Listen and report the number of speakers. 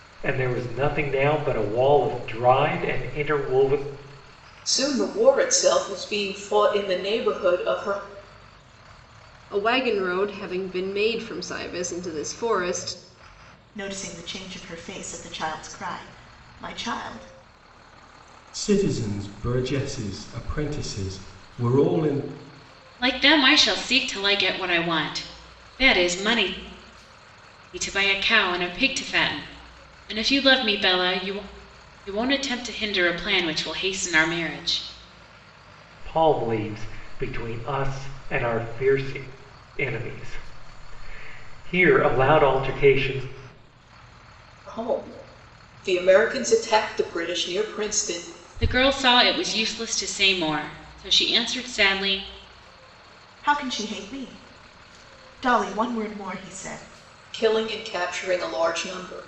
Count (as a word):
six